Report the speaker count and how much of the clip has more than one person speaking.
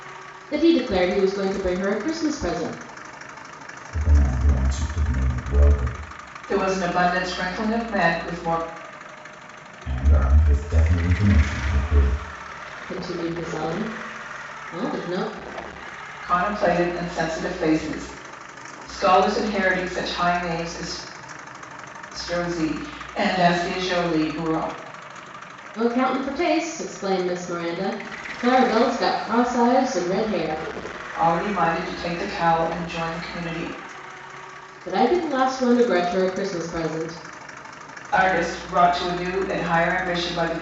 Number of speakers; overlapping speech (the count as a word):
three, no overlap